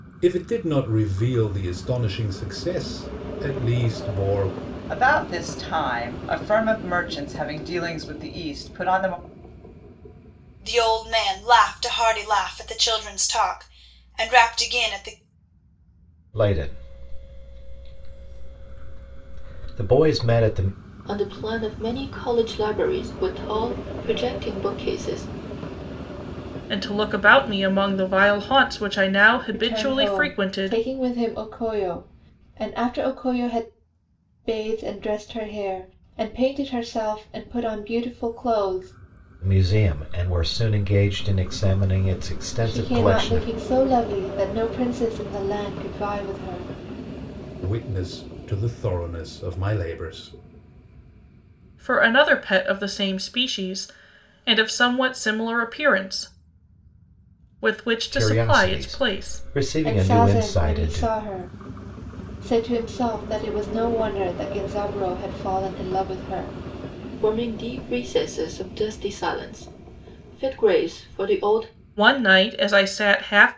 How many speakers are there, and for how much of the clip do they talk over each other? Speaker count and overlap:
seven, about 7%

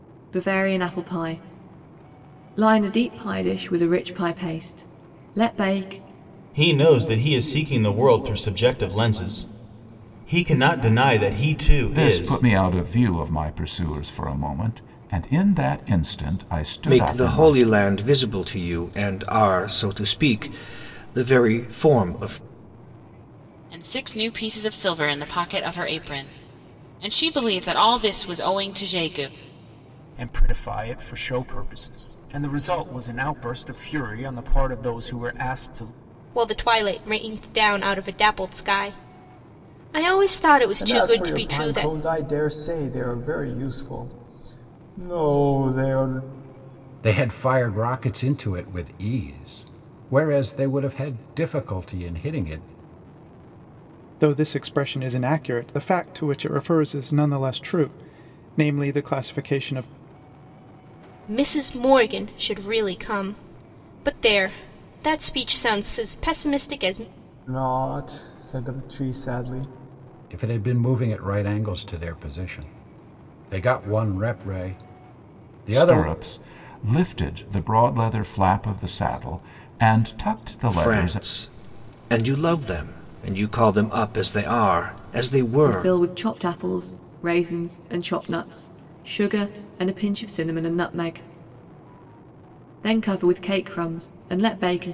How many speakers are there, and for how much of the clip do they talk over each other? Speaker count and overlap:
ten, about 4%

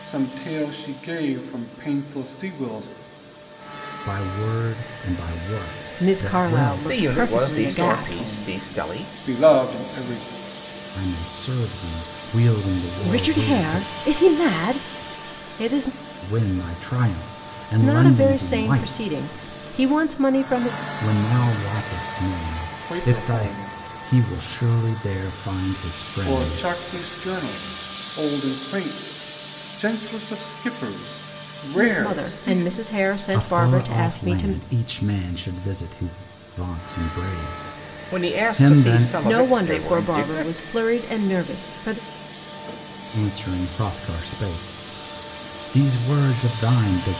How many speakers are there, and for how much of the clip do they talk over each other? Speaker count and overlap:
four, about 24%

